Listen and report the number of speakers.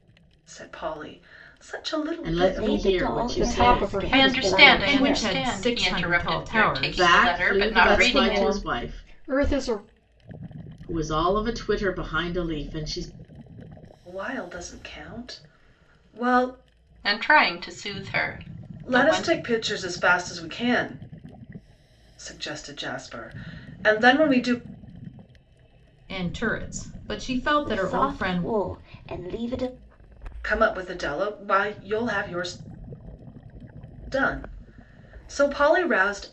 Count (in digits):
6